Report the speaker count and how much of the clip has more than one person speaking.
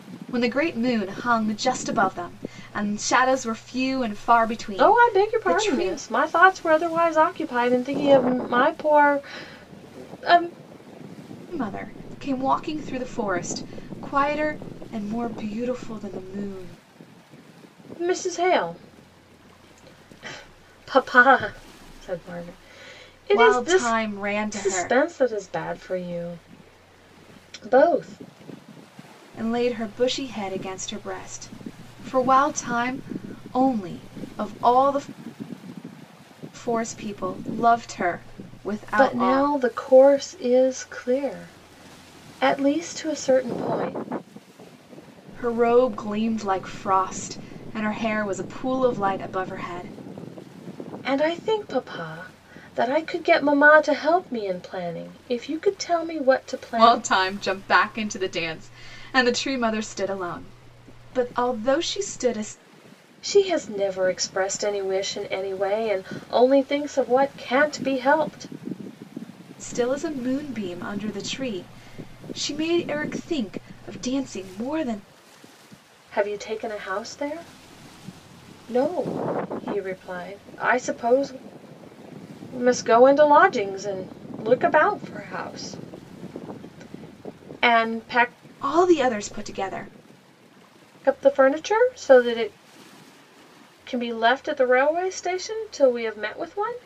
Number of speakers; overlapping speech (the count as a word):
two, about 3%